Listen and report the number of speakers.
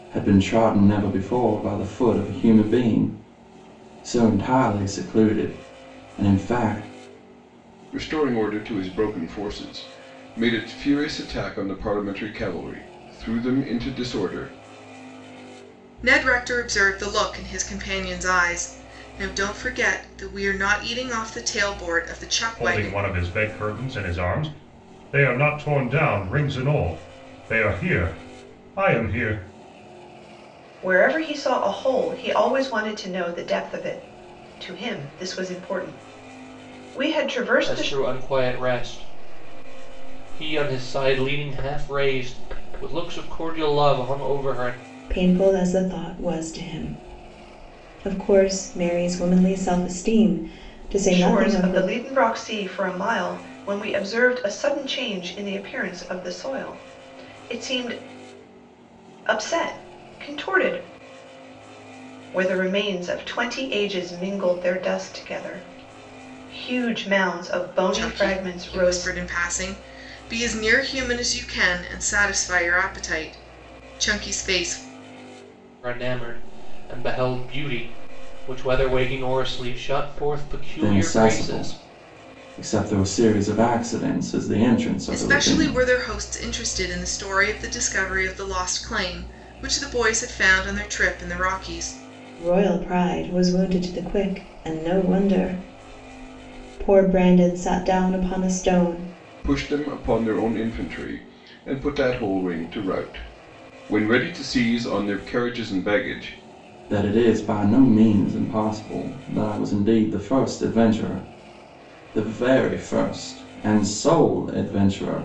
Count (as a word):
seven